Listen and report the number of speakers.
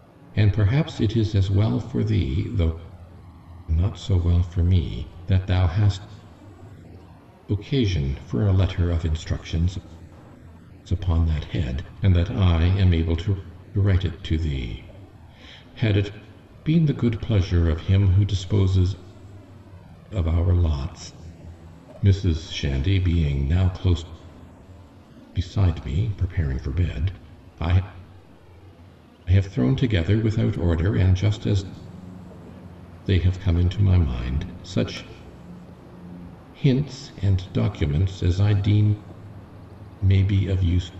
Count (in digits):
1